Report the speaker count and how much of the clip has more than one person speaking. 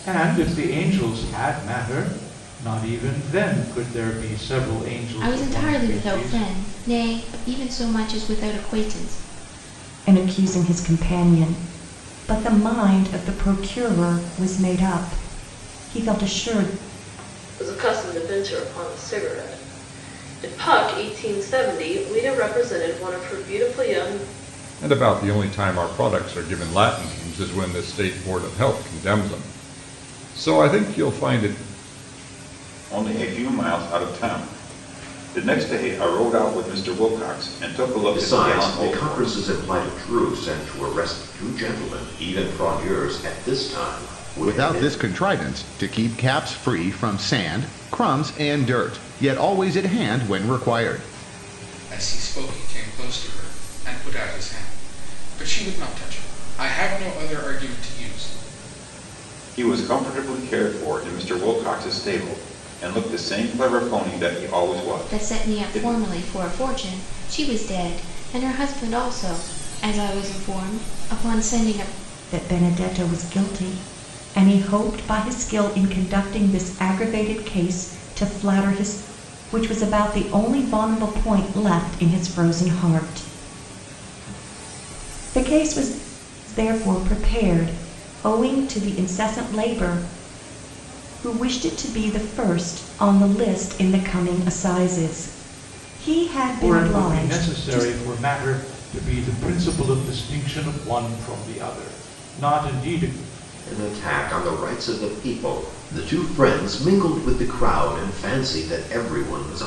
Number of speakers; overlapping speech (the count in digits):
9, about 5%